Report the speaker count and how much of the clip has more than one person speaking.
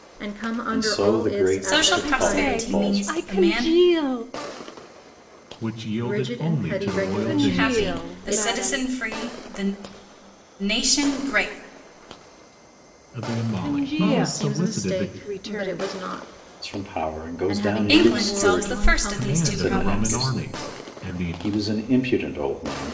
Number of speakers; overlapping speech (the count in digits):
5, about 53%